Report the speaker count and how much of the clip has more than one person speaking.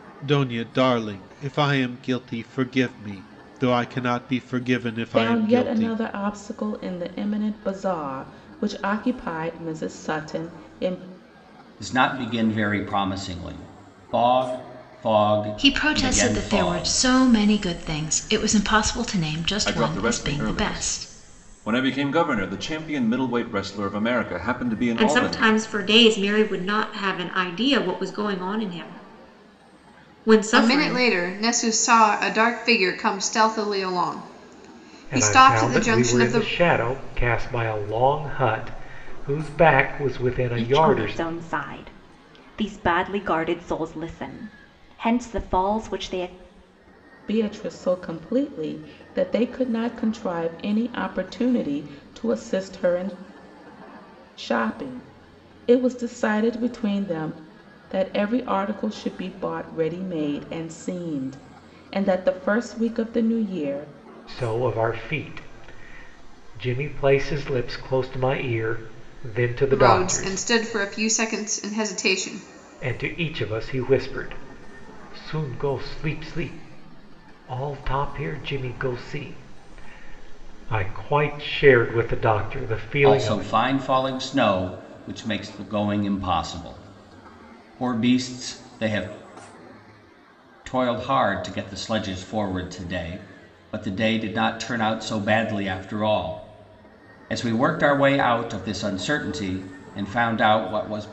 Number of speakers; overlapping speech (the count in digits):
9, about 8%